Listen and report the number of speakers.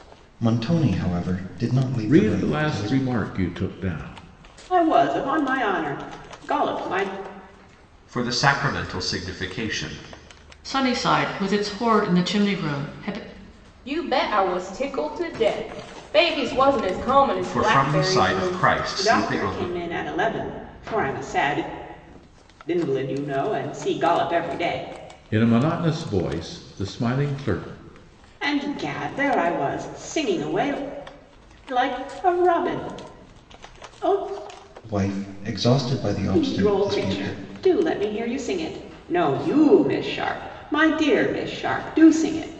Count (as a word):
six